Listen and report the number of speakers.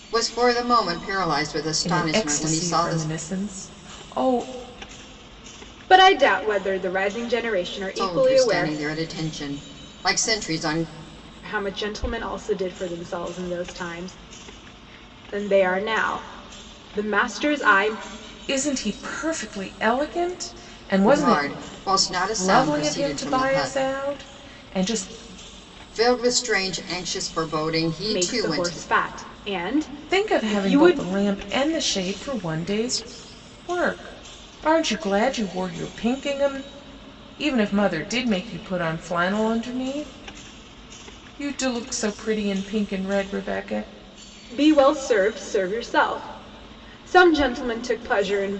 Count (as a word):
three